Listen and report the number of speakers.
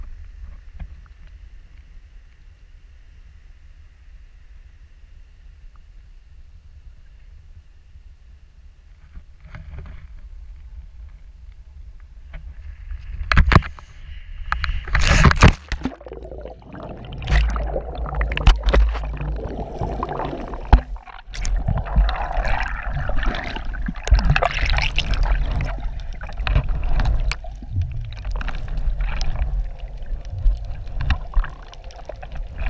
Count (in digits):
0